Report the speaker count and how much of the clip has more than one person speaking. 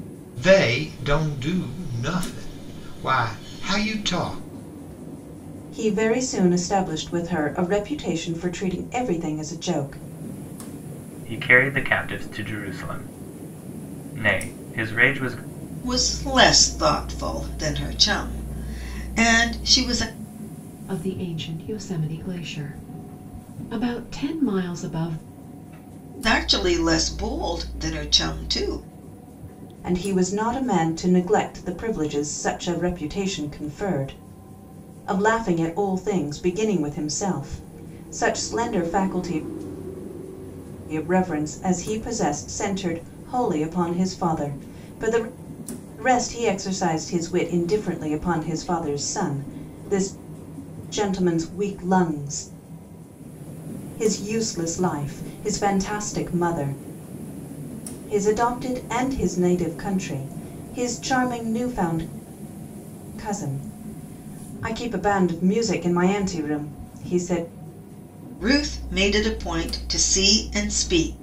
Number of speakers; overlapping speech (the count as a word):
five, no overlap